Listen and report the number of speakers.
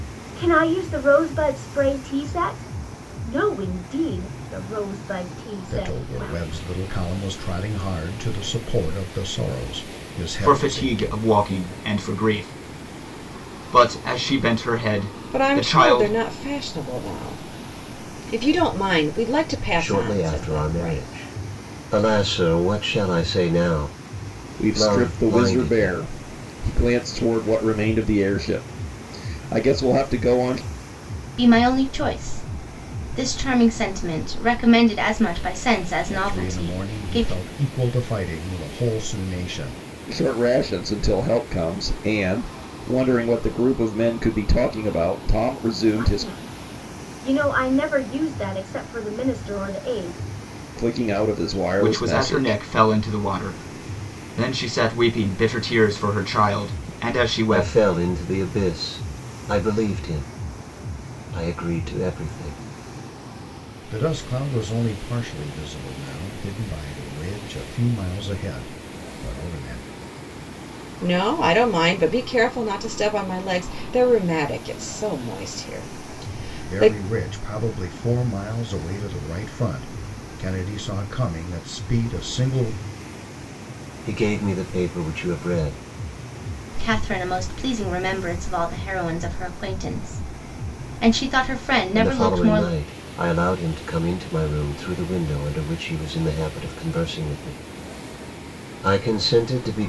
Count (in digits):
7